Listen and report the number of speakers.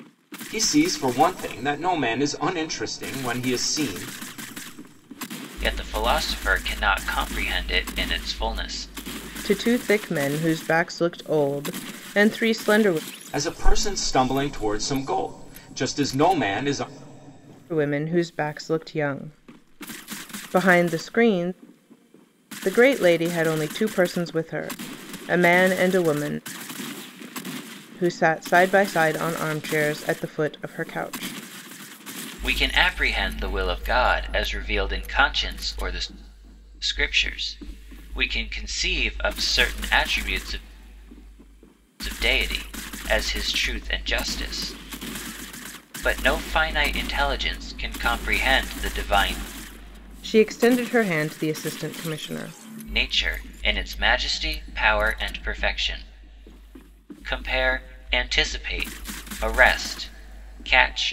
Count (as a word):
three